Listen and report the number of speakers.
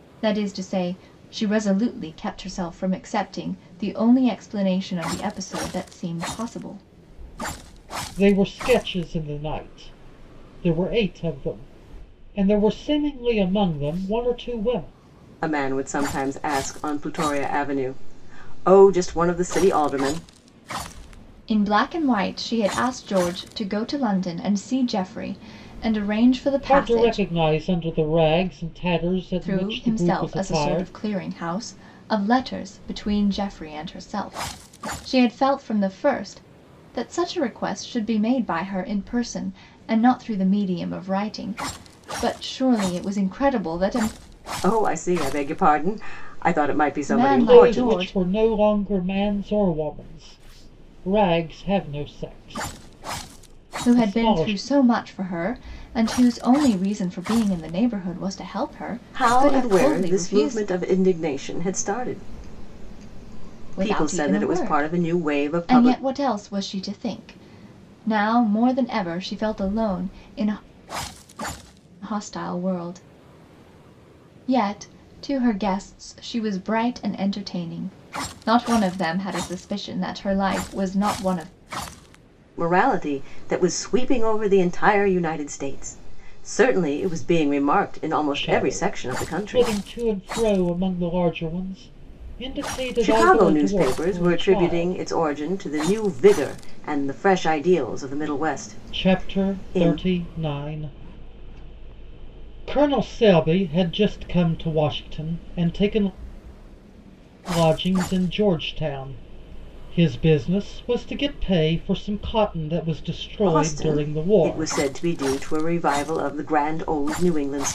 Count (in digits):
3